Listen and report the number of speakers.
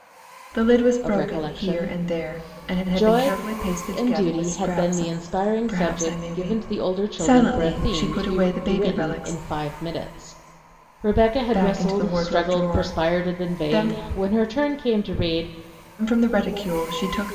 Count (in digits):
2